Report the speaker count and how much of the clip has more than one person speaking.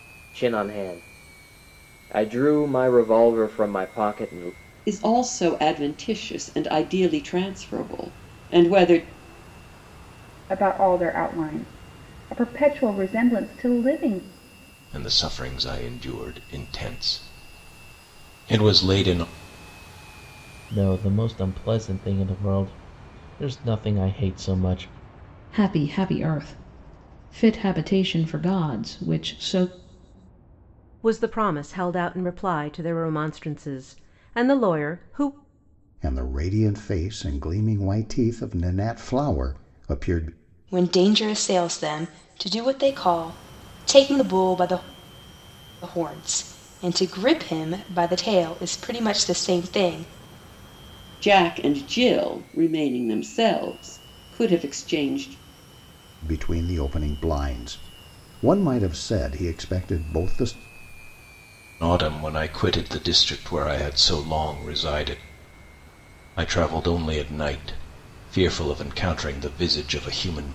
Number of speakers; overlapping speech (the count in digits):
9, no overlap